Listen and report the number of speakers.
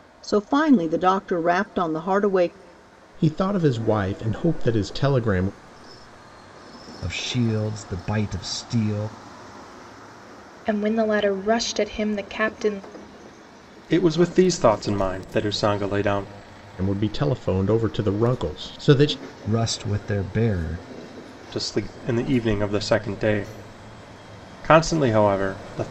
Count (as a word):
five